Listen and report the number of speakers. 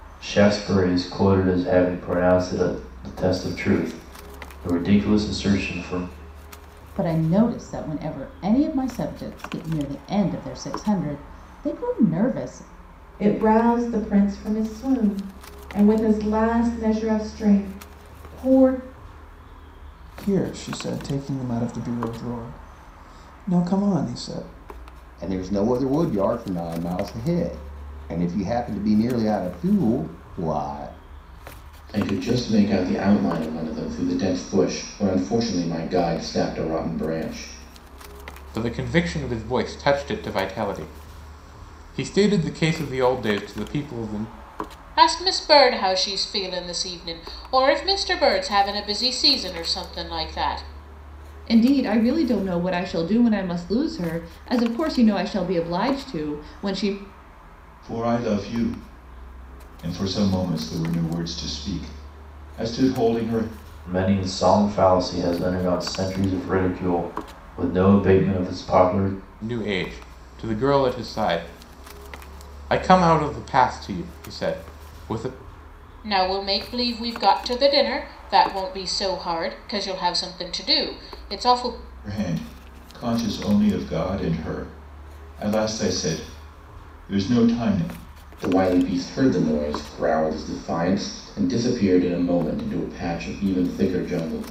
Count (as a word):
ten